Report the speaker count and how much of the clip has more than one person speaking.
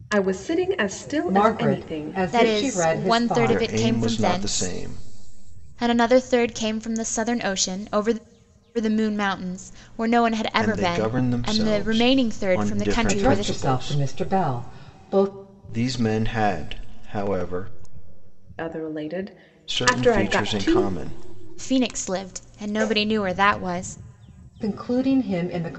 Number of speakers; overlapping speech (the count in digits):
4, about 30%